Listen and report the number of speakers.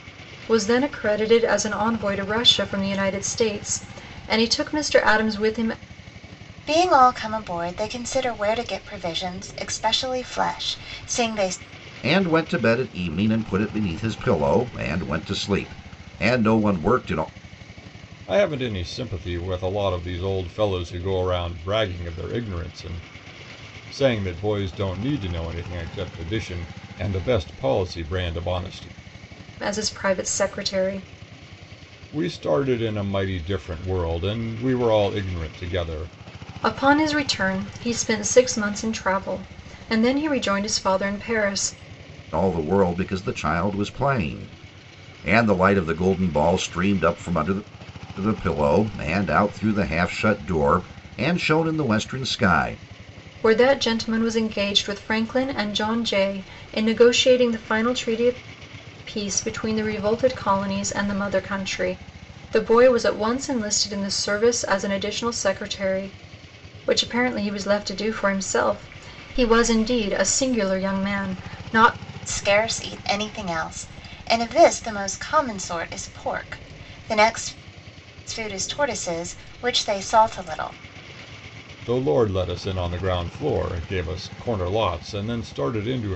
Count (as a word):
four